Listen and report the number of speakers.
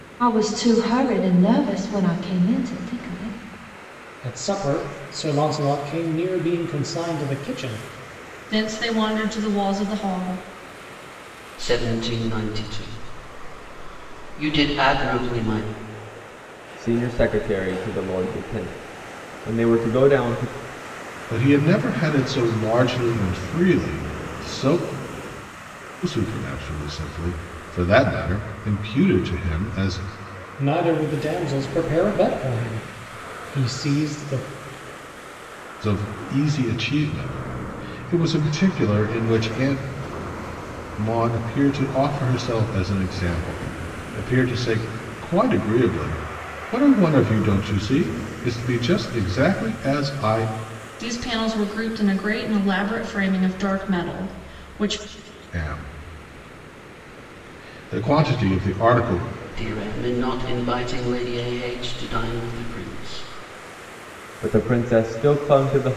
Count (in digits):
6